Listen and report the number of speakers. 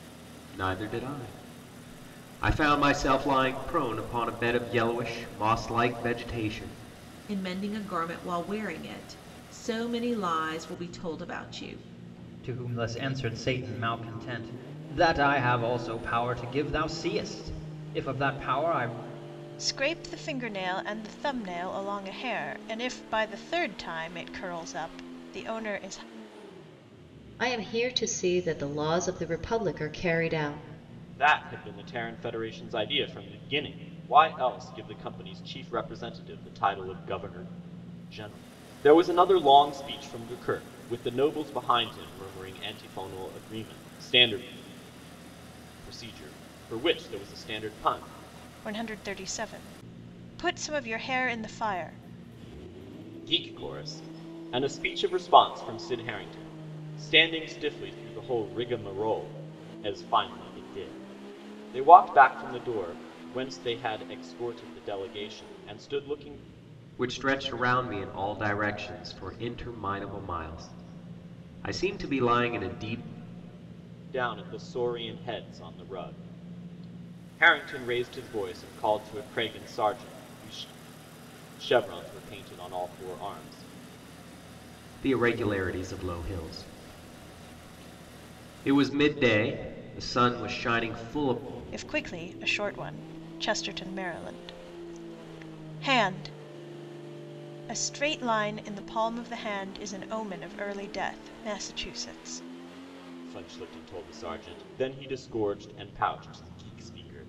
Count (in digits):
6